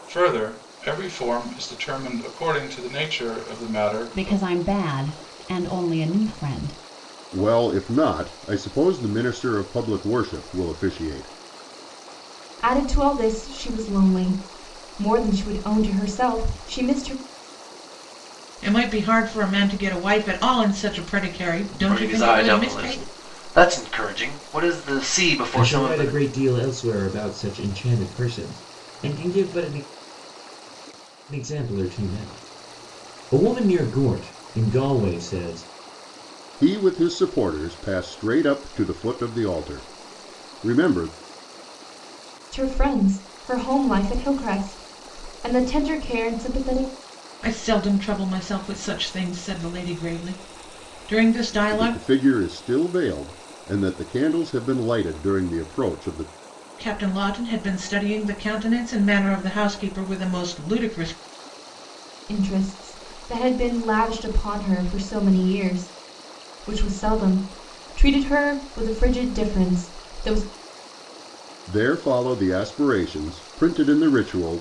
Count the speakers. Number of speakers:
seven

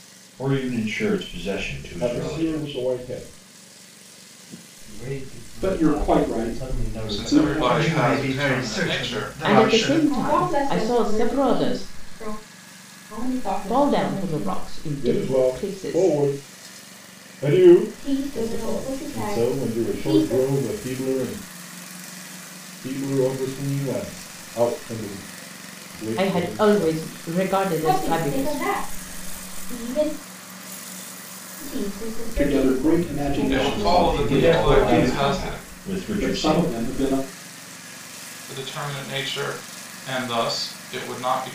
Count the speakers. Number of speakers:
eight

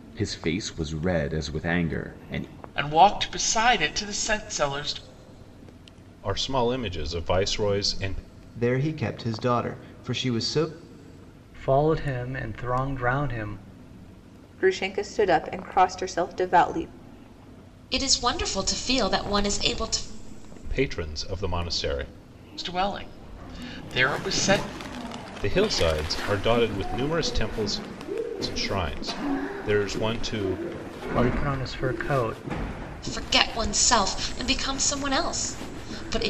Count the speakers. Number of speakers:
seven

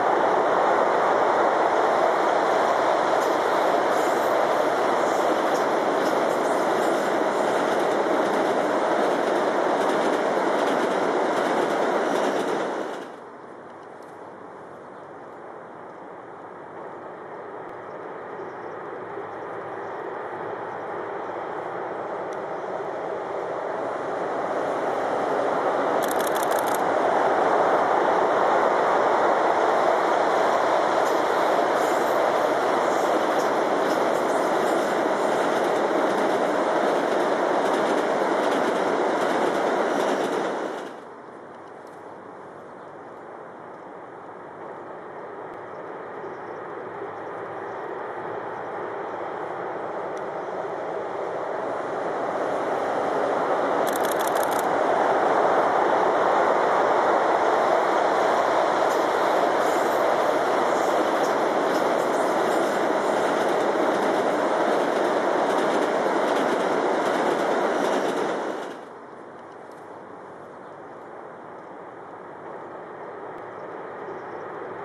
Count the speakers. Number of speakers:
zero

